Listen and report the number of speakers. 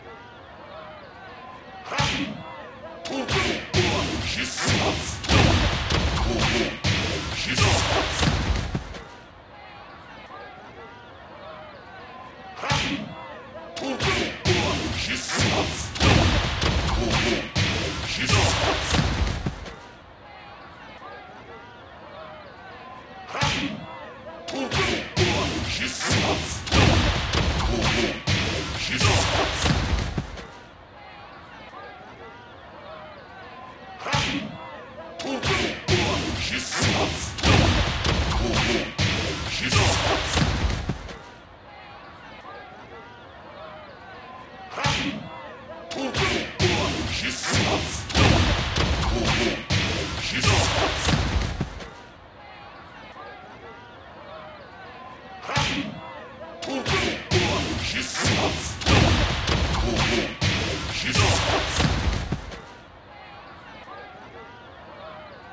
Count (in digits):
0